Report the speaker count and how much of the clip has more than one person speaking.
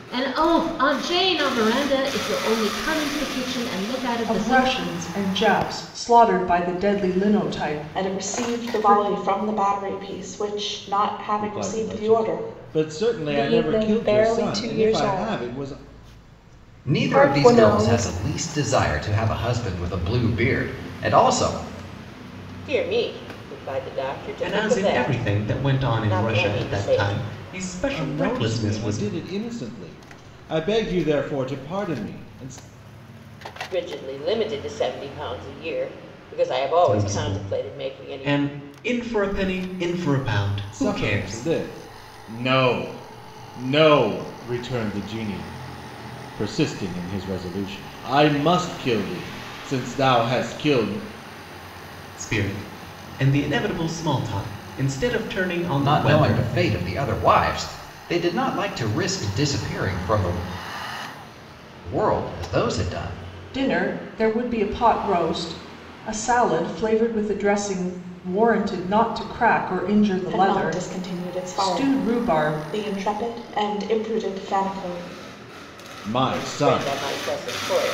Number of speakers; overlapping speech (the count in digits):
8, about 22%